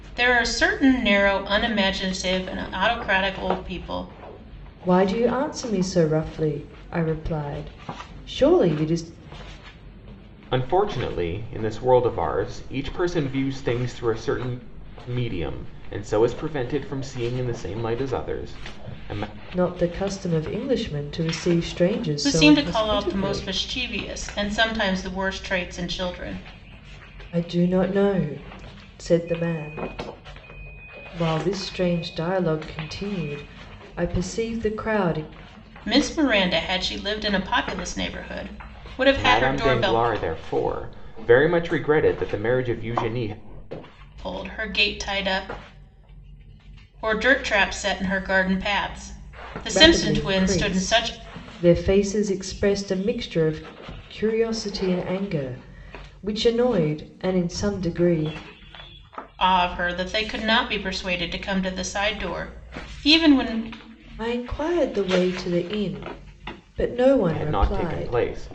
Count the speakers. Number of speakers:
three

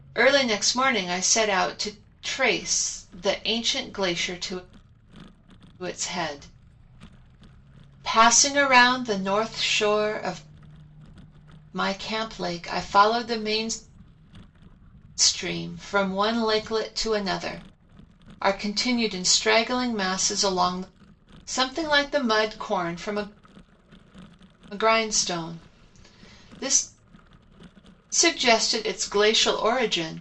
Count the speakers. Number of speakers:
one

